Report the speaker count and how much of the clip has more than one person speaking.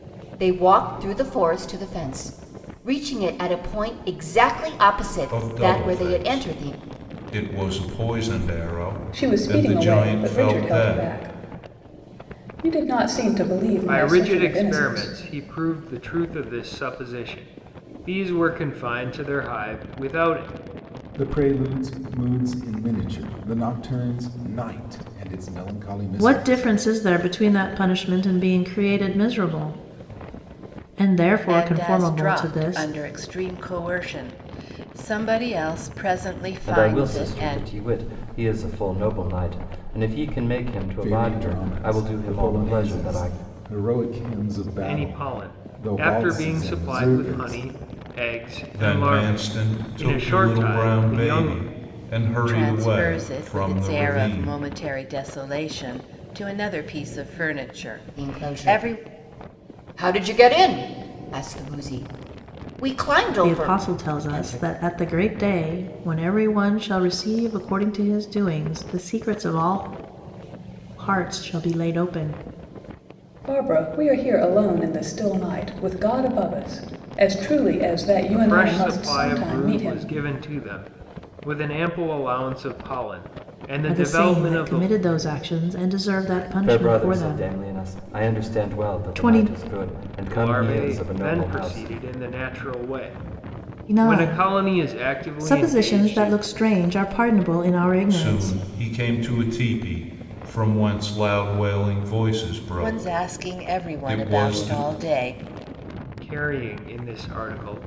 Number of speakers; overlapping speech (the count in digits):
8, about 31%